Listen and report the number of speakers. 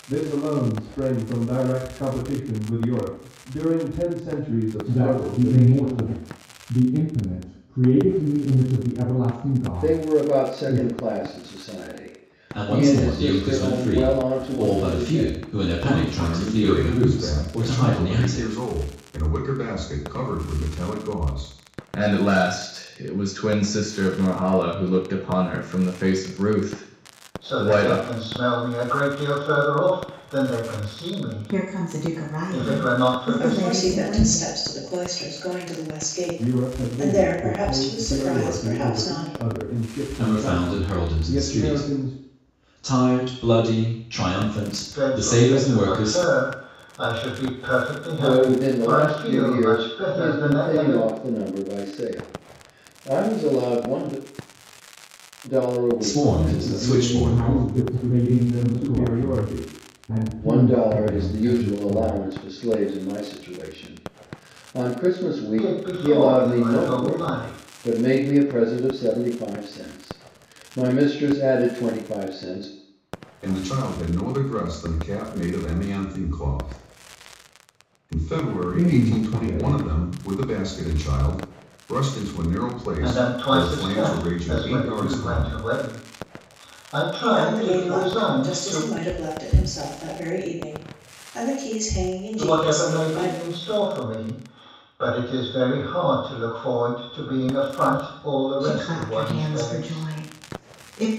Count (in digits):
9